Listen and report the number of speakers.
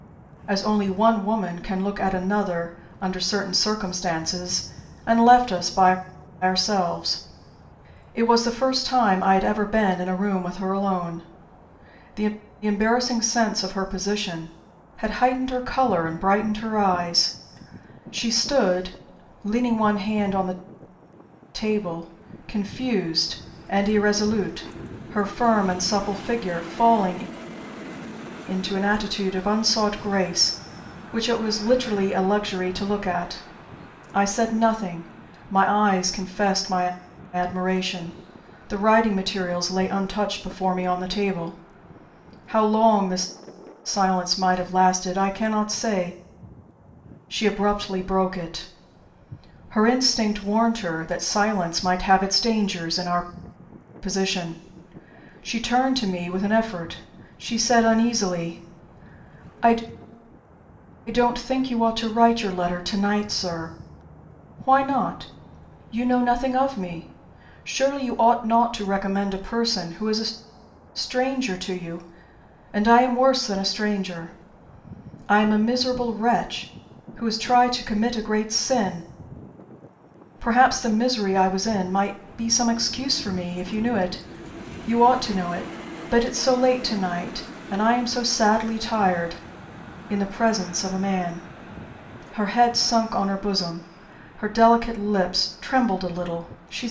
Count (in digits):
1